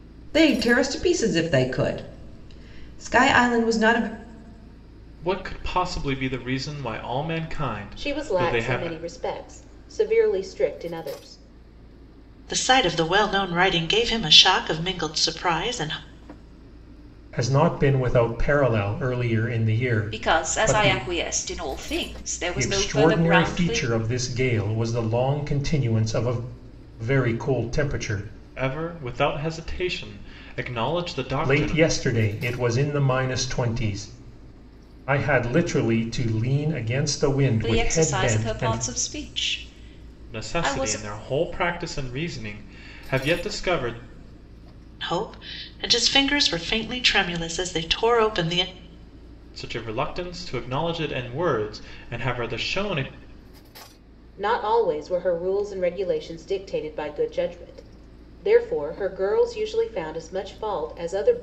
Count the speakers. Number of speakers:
six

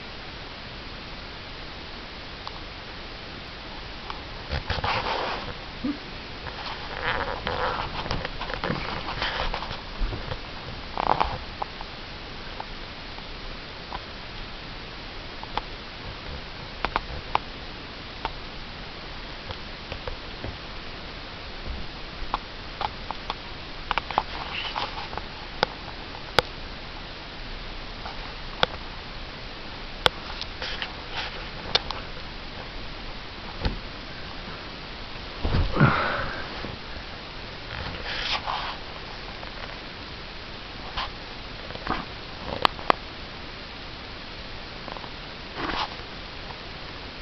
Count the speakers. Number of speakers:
zero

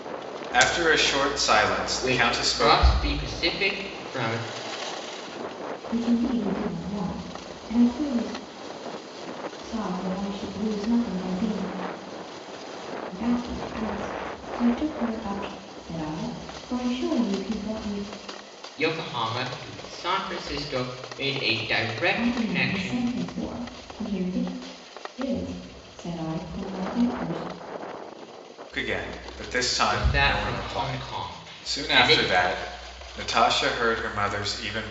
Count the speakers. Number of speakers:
three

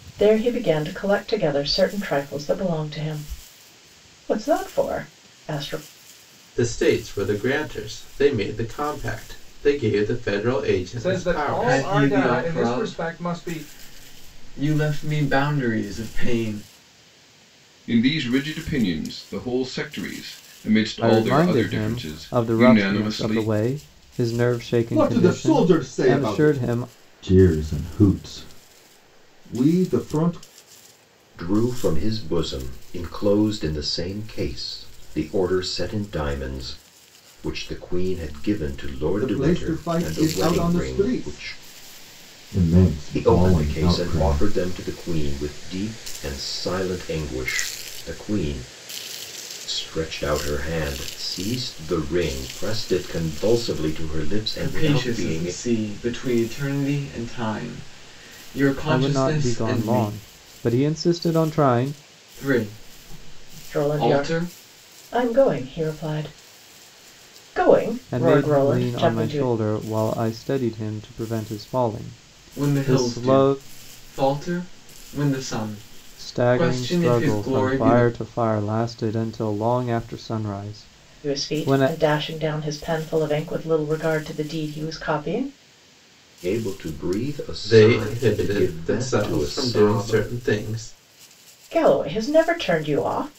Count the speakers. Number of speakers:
eight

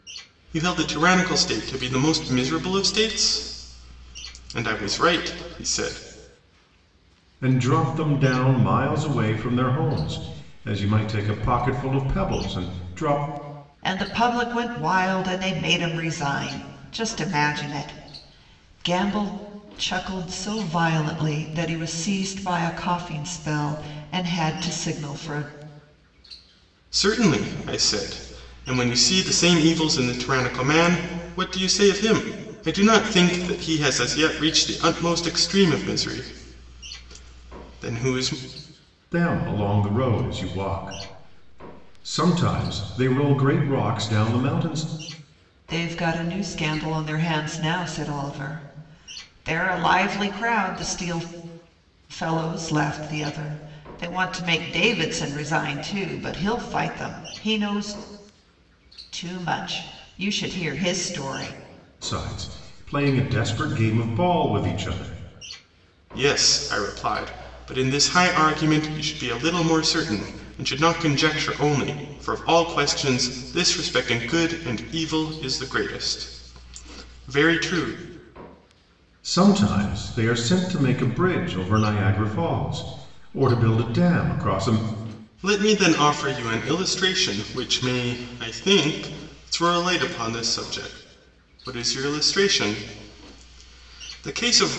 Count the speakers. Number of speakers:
three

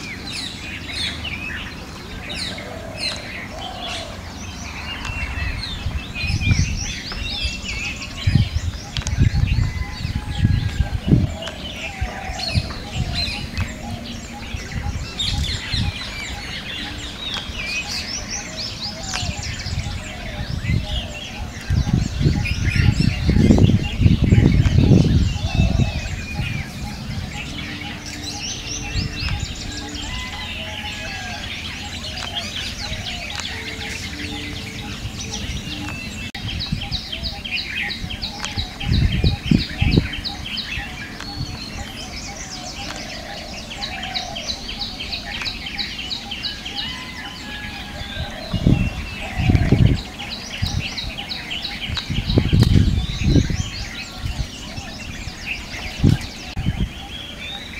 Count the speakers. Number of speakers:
zero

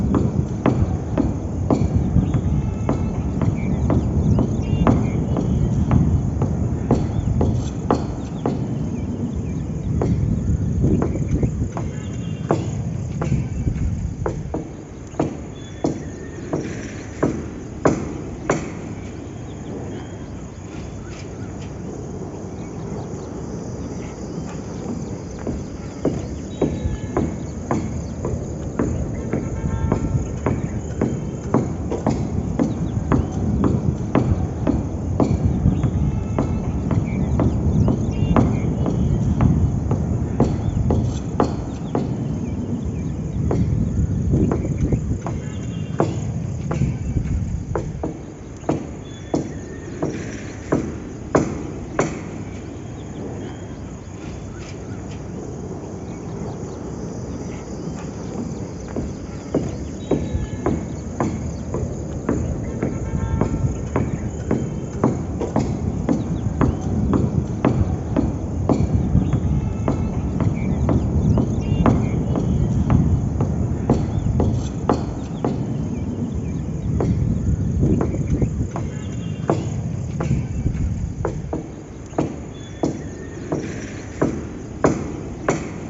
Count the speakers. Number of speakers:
zero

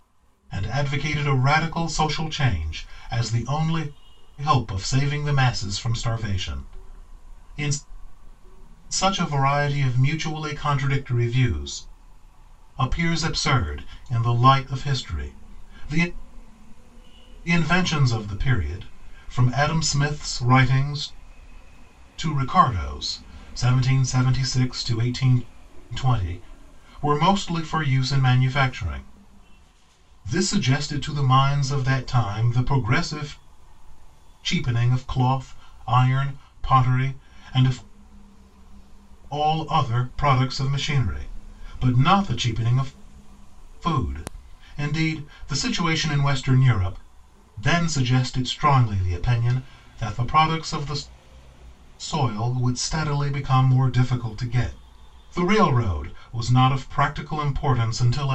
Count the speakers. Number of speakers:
one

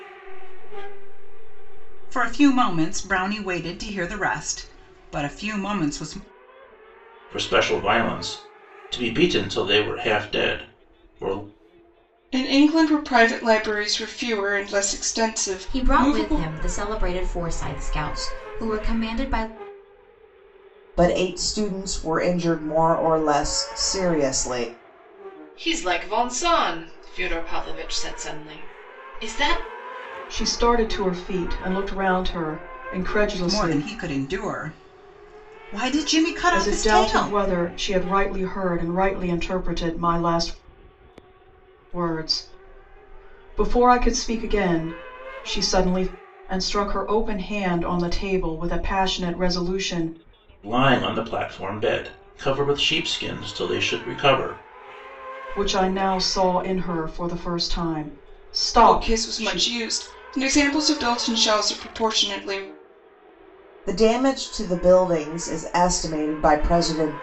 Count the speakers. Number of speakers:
eight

